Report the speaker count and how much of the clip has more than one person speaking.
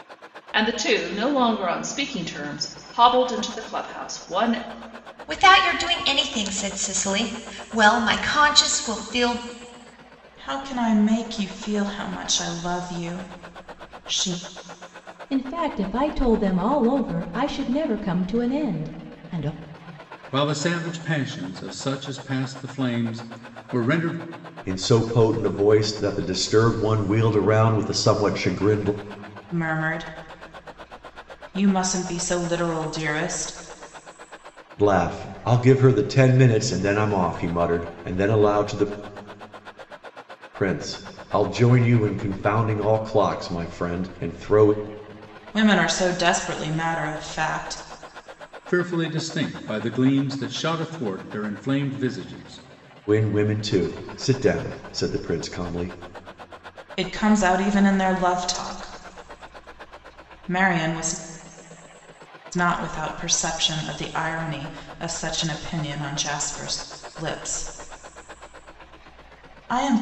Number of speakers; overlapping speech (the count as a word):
six, no overlap